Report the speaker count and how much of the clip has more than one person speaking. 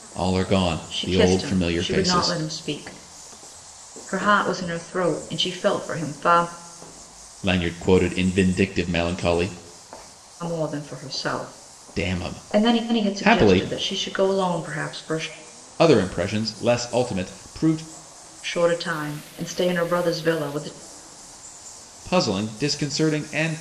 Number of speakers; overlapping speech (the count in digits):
2, about 14%